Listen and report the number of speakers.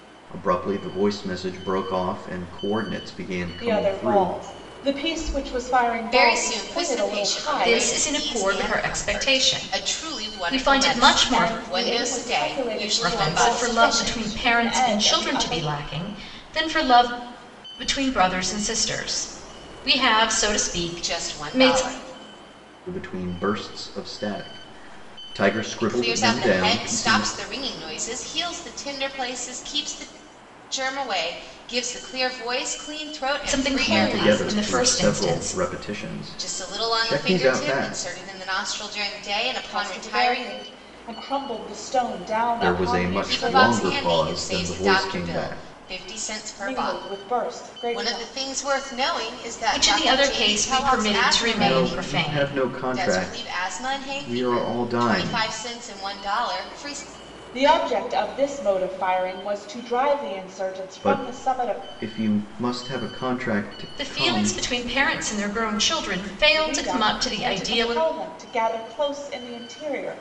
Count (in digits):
4